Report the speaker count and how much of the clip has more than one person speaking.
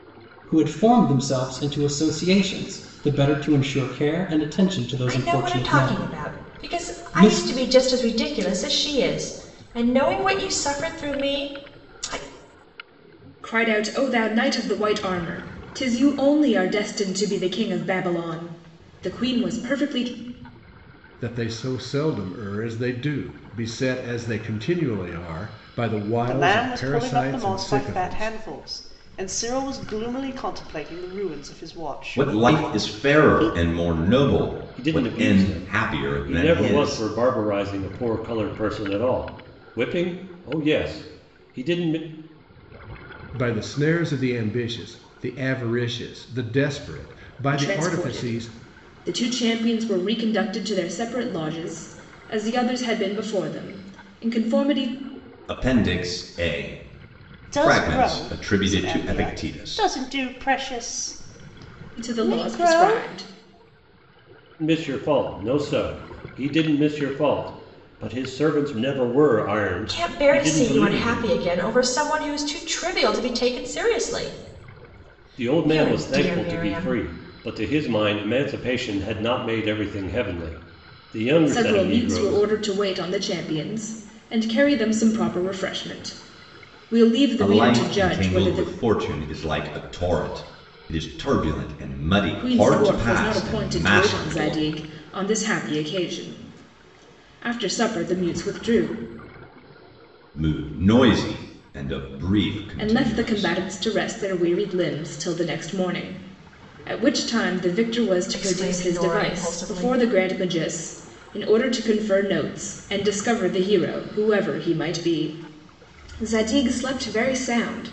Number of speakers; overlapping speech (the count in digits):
7, about 20%